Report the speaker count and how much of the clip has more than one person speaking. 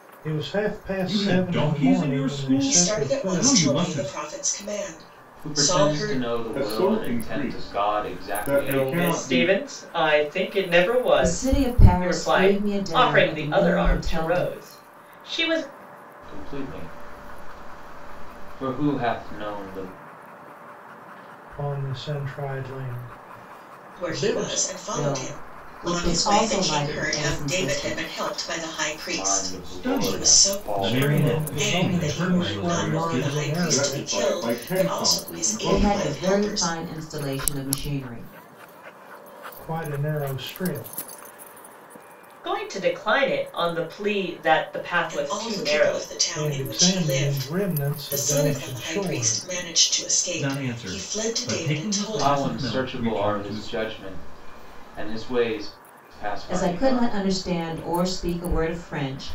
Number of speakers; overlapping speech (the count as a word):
seven, about 50%